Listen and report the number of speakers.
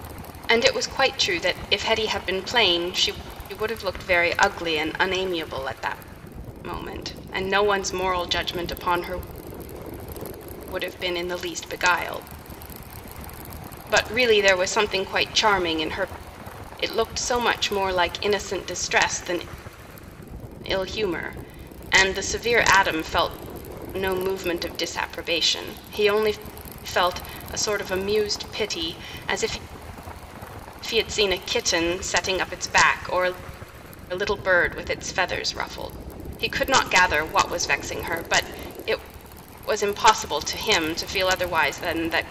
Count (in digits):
1